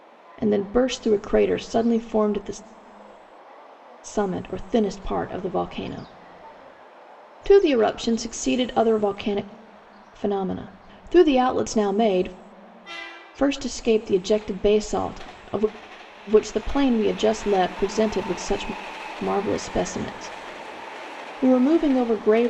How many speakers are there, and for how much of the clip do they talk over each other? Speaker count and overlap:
one, no overlap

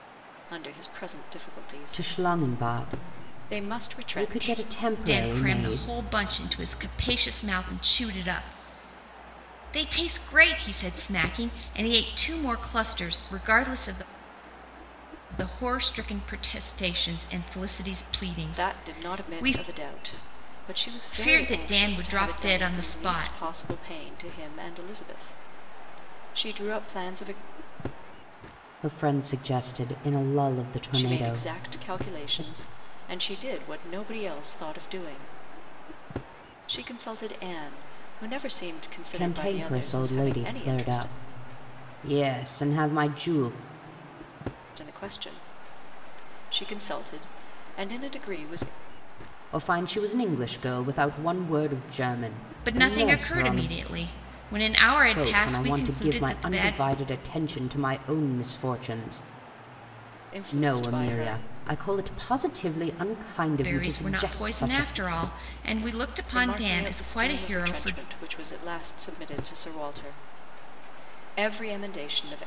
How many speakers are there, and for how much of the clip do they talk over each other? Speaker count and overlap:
three, about 24%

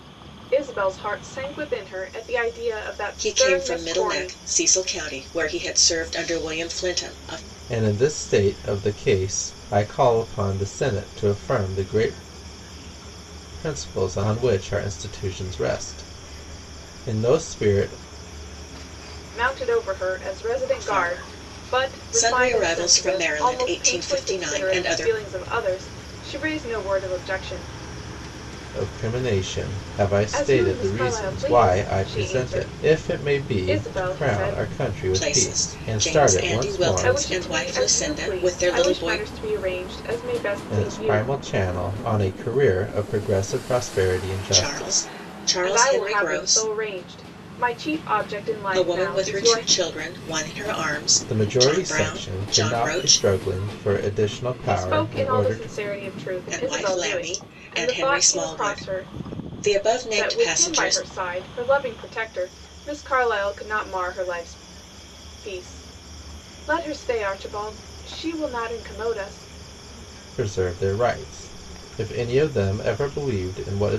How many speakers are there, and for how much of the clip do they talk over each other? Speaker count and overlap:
three, about 33%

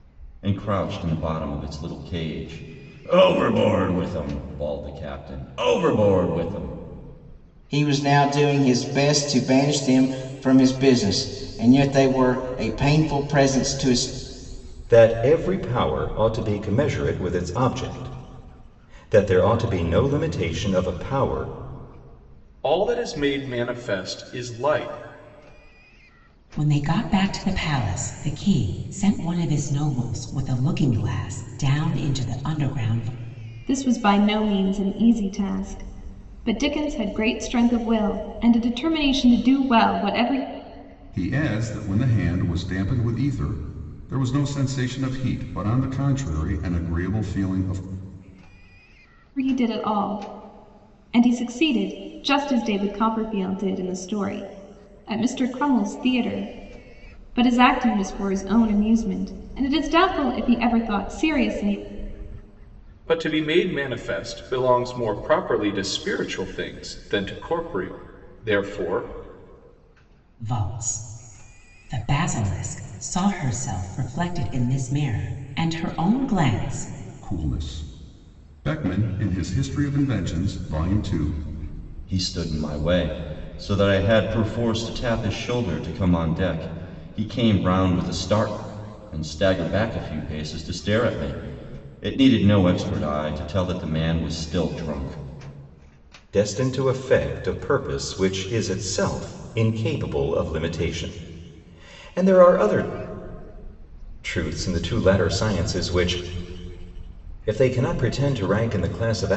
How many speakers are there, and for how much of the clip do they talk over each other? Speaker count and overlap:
seven, no overlap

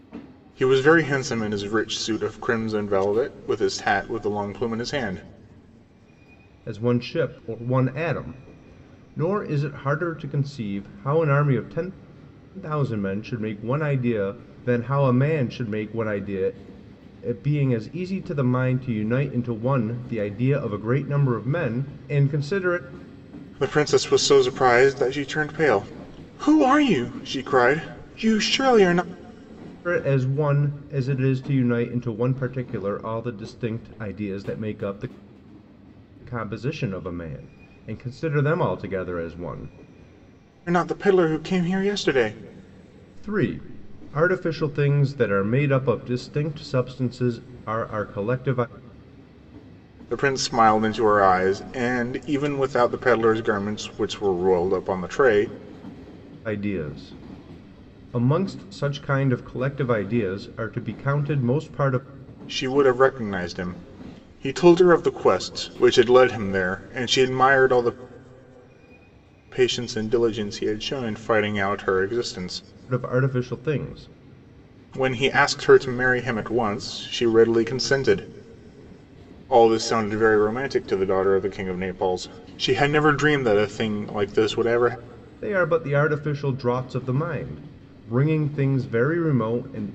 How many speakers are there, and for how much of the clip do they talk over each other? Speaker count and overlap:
two, no overlap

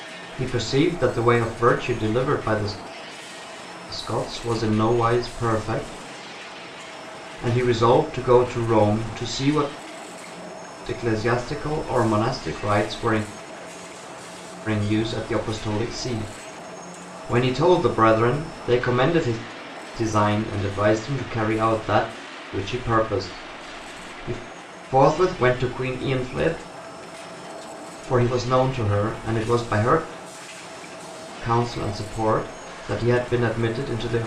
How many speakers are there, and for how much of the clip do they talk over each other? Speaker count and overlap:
one, no overlap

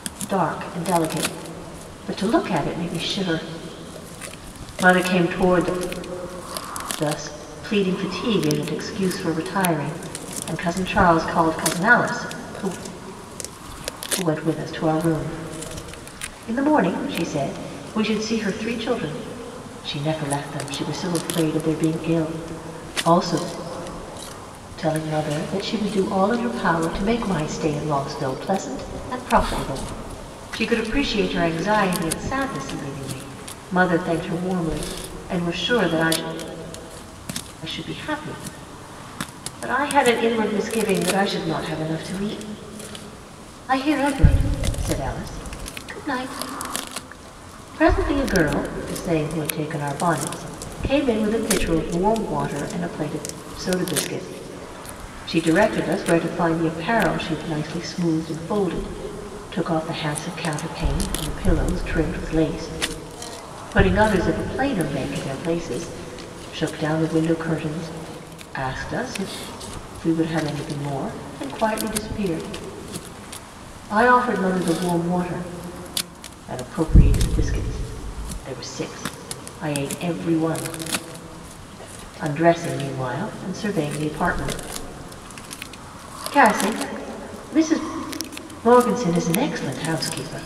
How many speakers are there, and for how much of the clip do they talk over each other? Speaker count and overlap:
one, no overlap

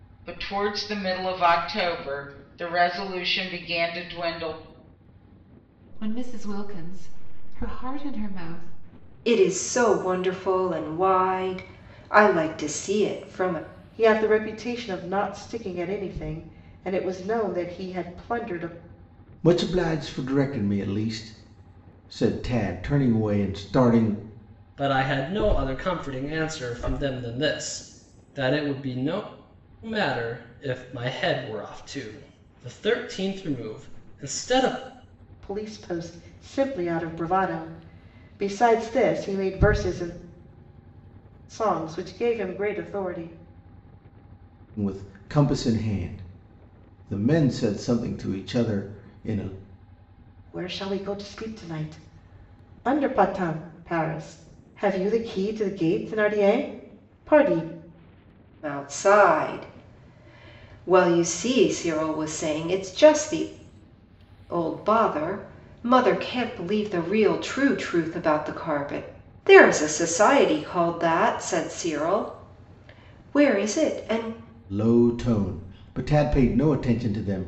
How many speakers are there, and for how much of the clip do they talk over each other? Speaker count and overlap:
six, no overlap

